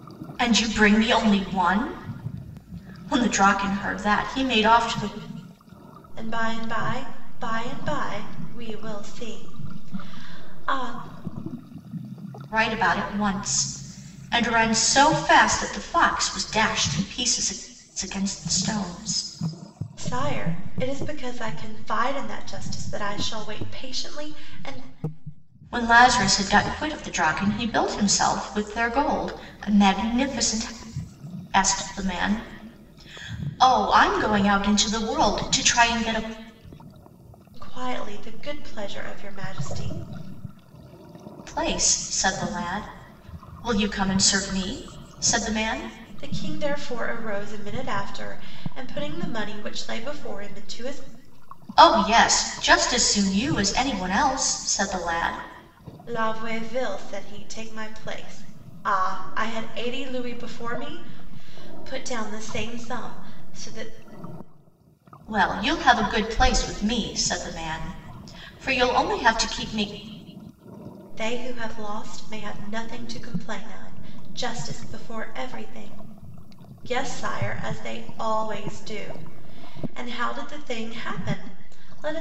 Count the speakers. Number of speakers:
two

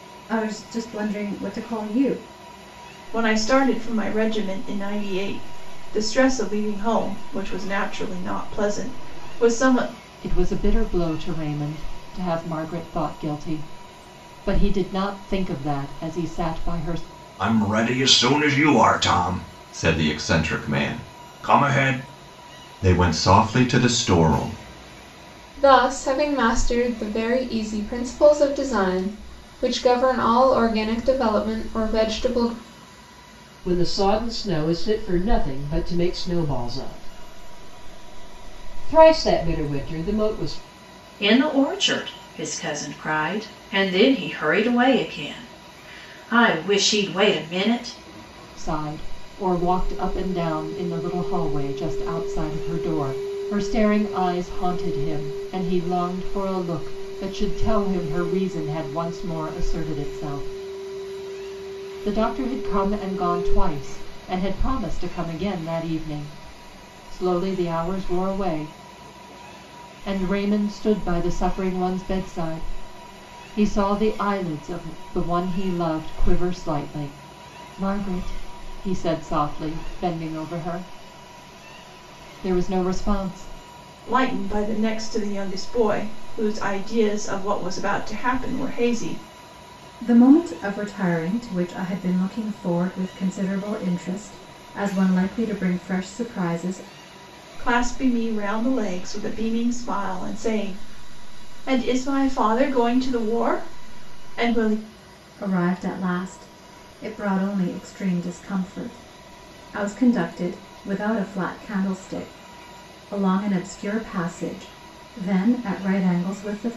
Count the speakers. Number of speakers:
seven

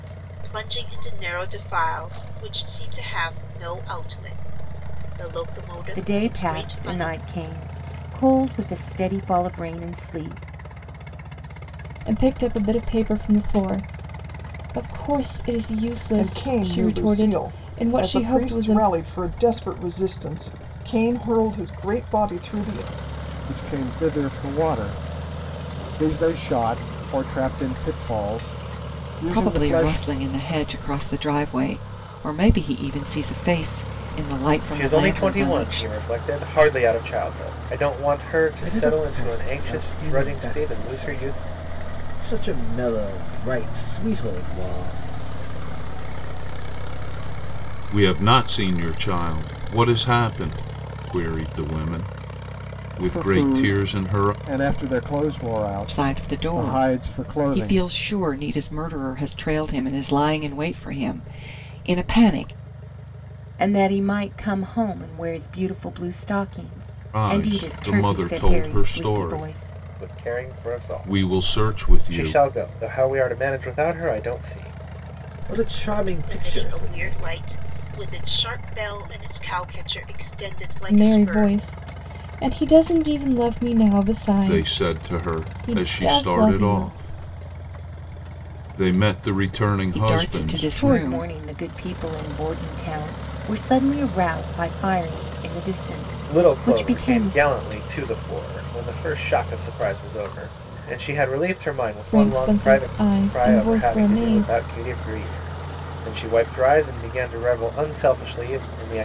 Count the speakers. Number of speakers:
ten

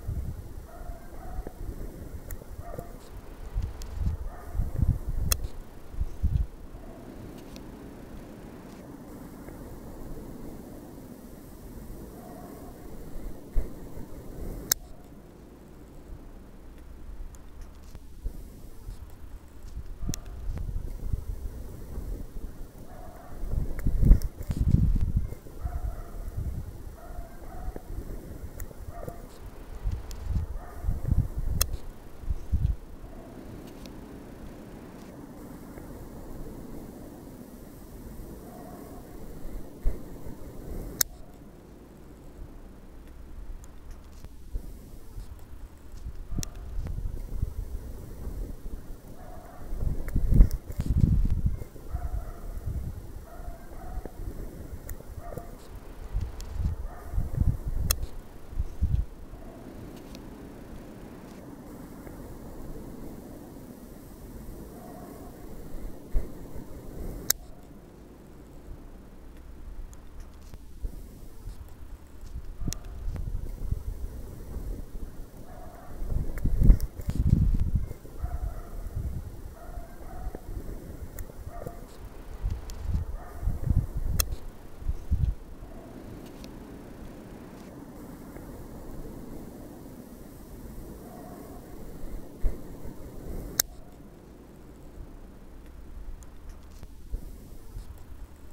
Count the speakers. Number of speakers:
zero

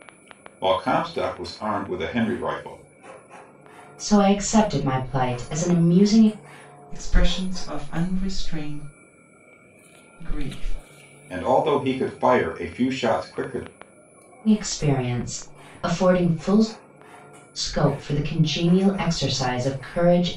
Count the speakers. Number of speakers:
three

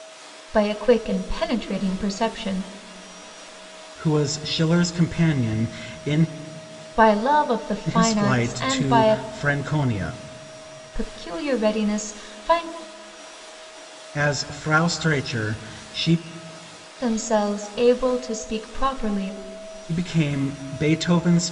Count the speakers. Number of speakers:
two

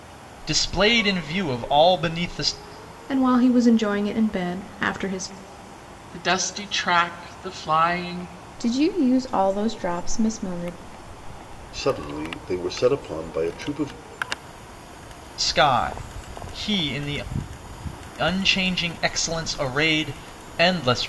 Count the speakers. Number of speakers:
five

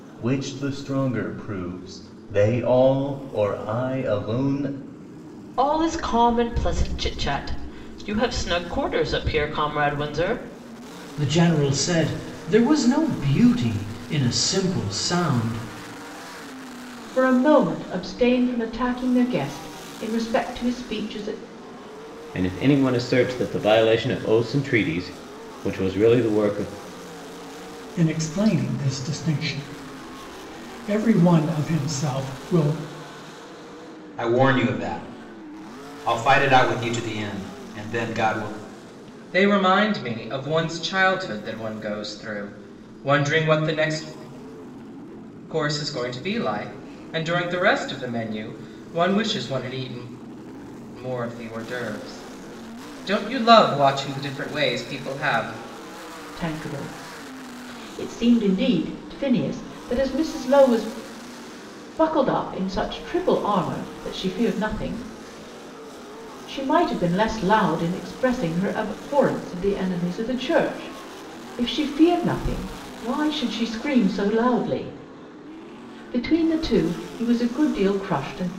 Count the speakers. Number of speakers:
eight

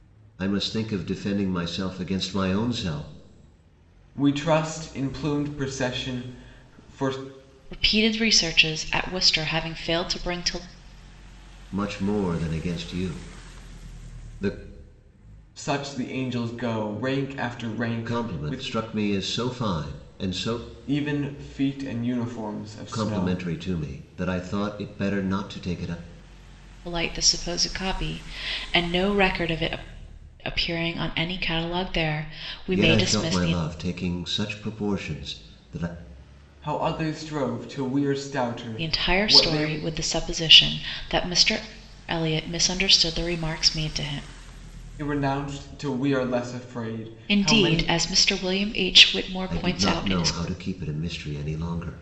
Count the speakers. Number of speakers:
three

